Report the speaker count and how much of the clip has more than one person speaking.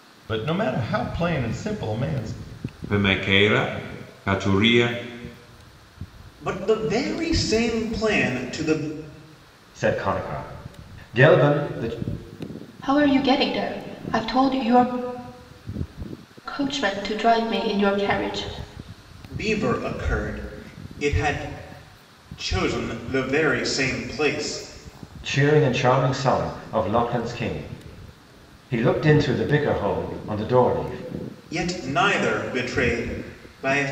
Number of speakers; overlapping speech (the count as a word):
five, no overlap